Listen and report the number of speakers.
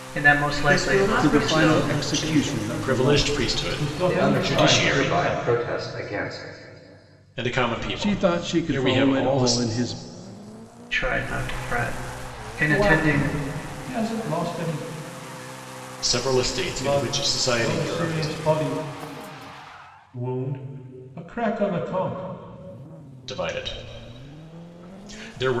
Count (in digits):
6